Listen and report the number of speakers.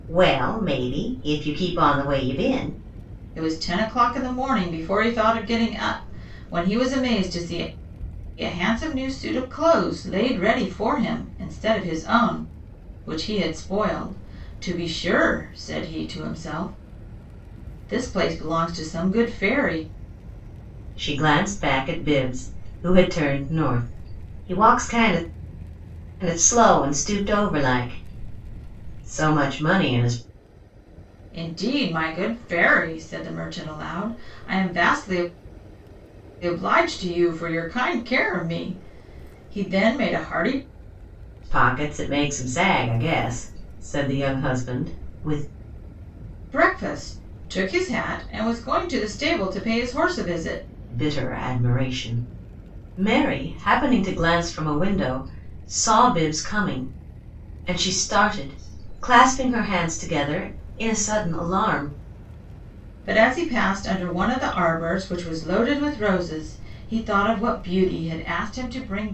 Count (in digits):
2